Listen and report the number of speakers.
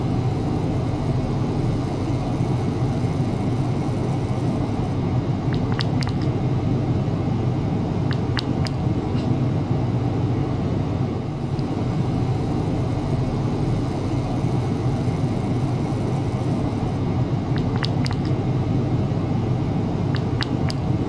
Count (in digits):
0